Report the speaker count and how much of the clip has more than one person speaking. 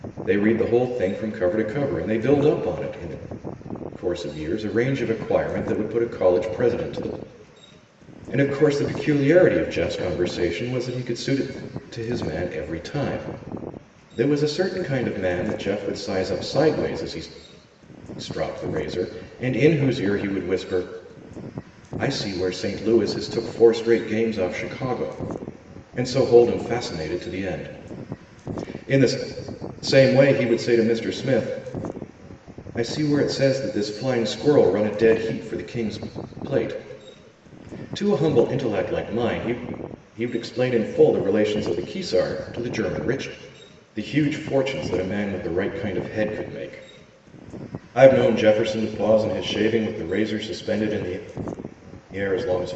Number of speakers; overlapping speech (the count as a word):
one, no overlap